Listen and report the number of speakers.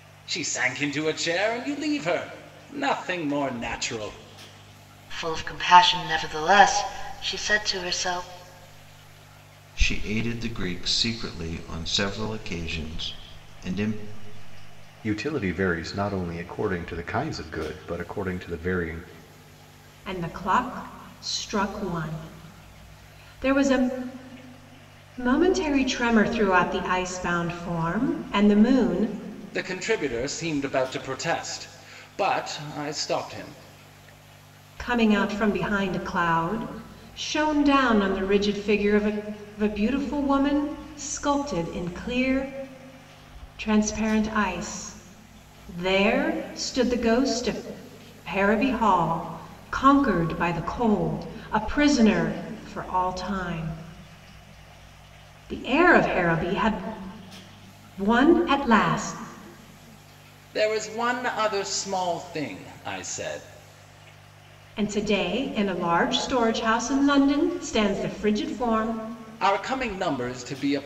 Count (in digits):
5